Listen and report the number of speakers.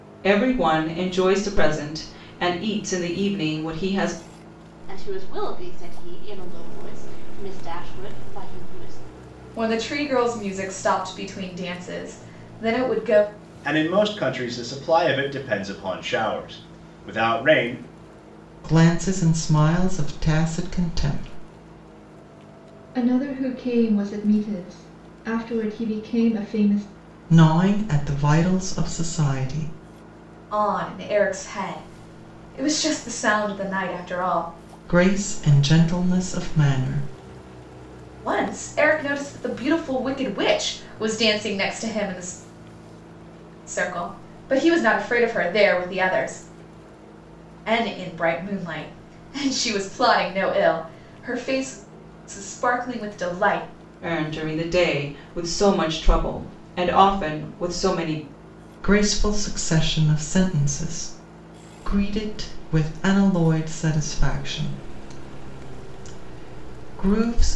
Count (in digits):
6